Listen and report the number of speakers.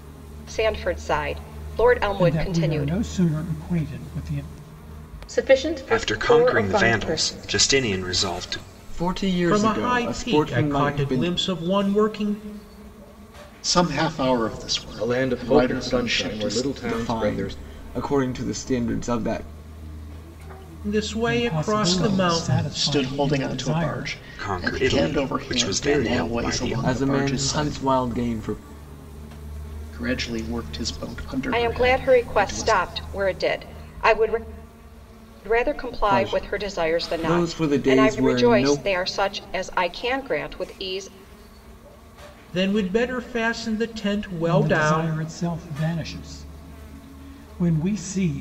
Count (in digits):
8